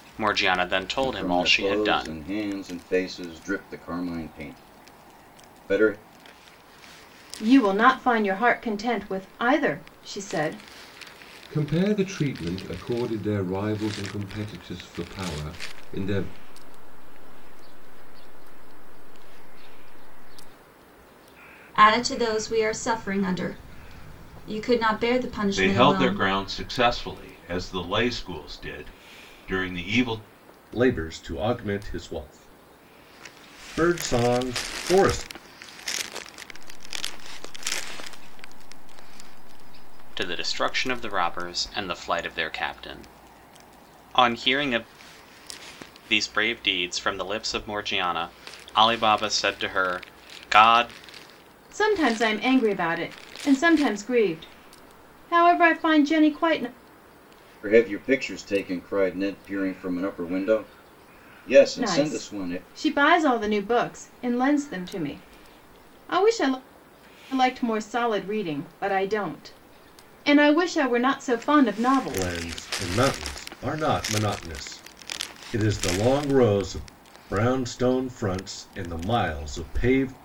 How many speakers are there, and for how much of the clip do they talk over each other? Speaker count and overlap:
8, about 7%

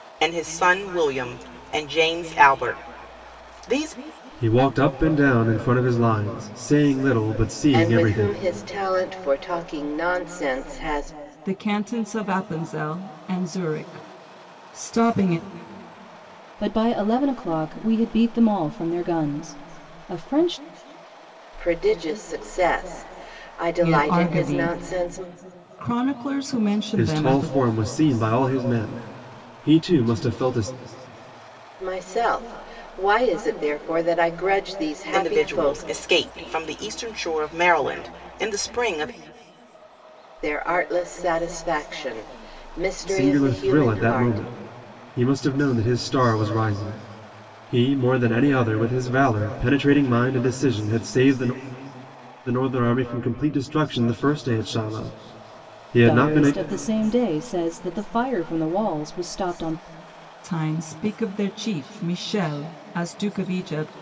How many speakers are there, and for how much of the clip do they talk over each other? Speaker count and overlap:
5, about 9%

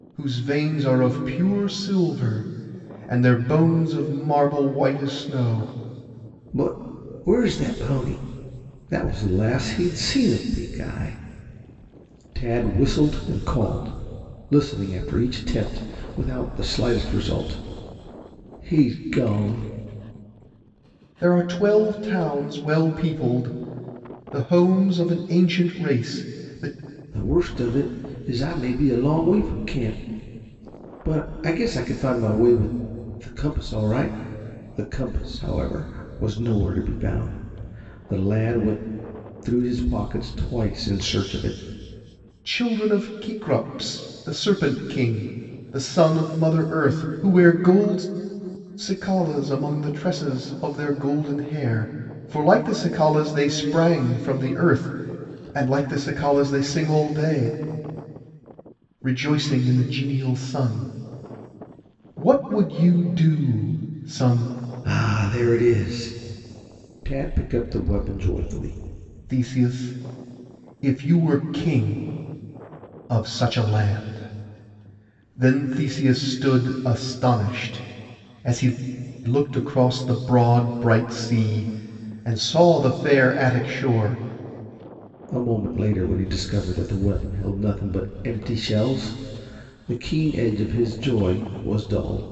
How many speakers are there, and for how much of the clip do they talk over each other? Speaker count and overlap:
2, no overlap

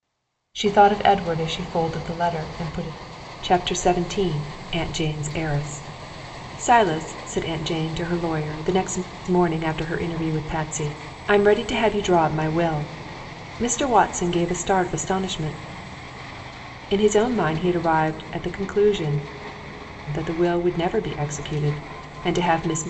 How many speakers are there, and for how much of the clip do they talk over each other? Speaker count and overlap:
1, no overlap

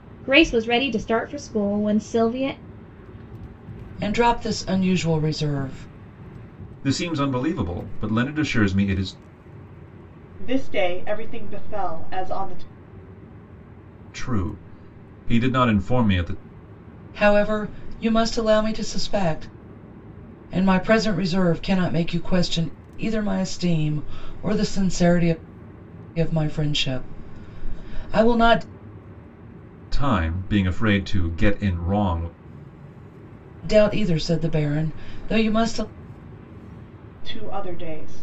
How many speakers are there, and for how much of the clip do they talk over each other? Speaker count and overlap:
4, no overlap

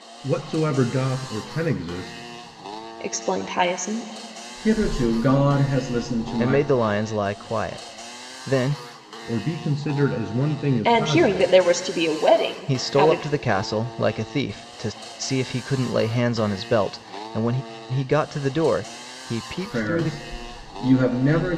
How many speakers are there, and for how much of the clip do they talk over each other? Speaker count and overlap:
4, about 11%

